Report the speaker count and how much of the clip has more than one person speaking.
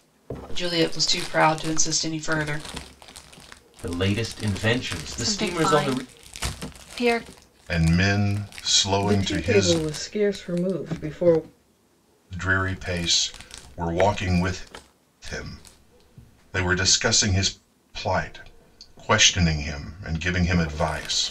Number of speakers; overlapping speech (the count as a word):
five, about 8%